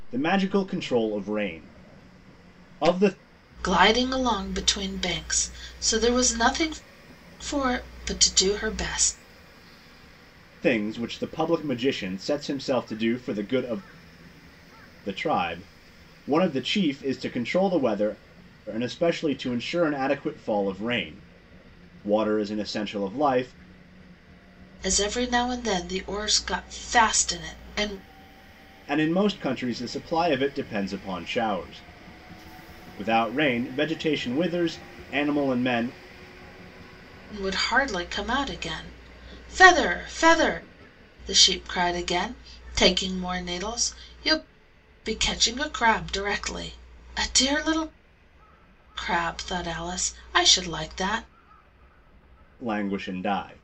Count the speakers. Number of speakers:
2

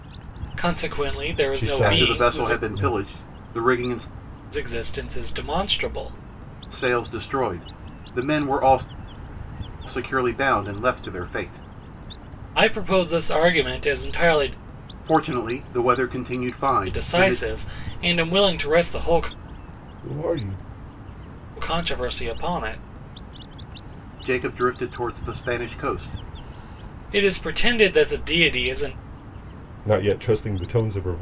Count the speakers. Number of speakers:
3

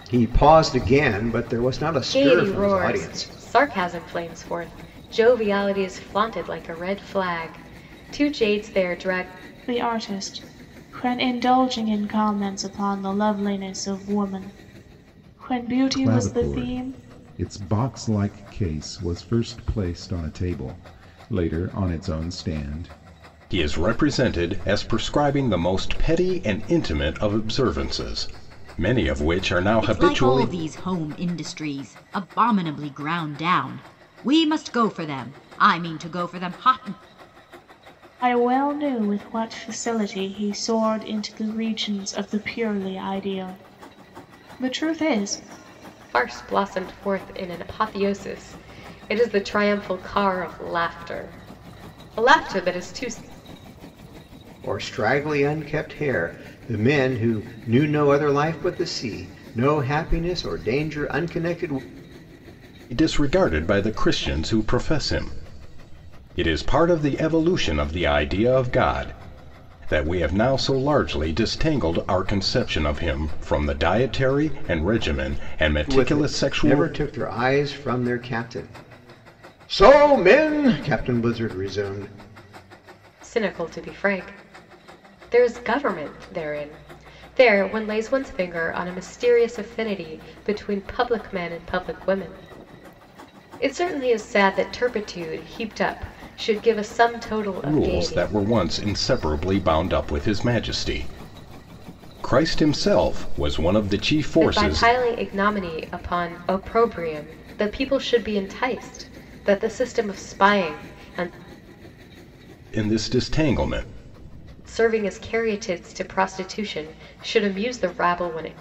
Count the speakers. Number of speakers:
6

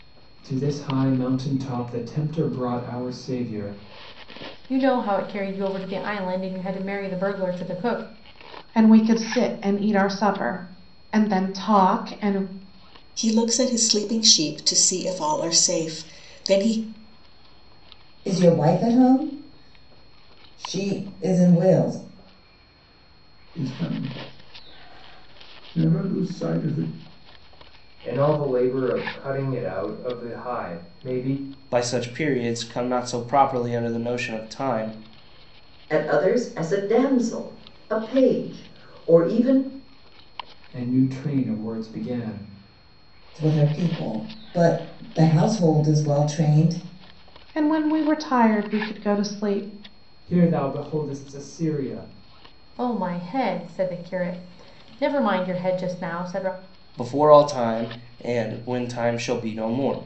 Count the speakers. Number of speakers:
9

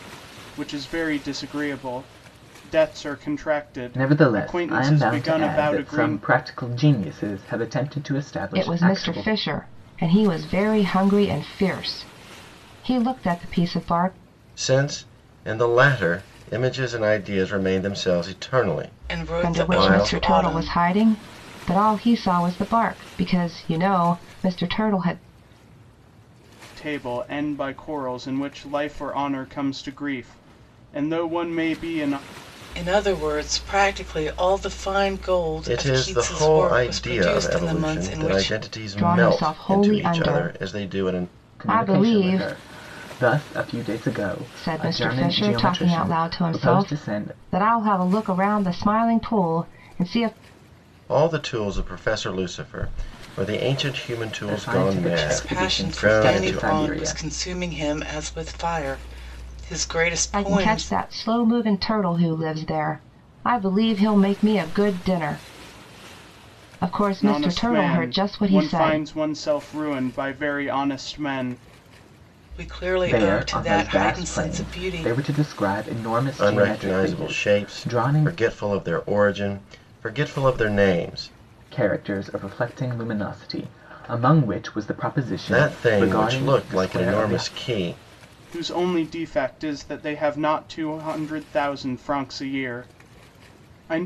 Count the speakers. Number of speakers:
5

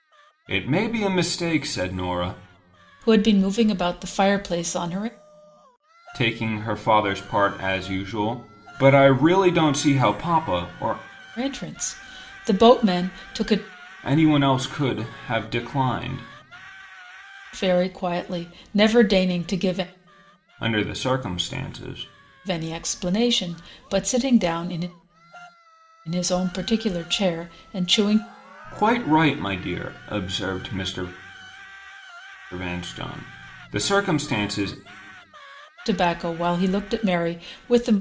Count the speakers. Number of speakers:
2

